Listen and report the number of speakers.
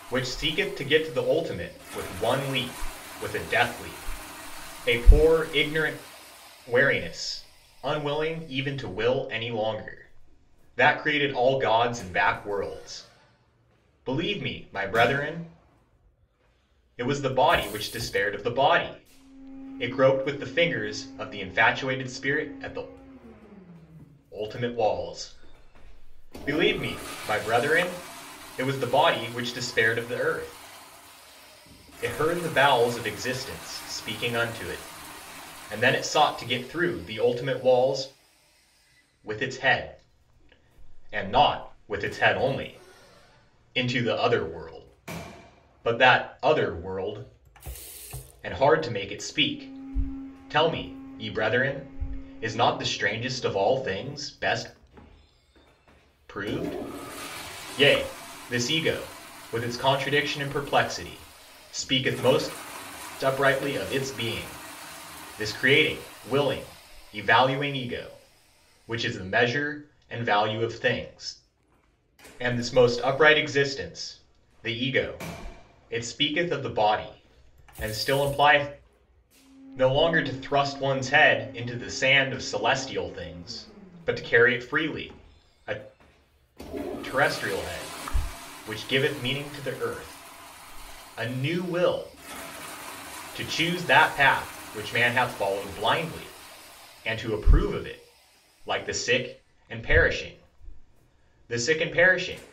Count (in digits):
1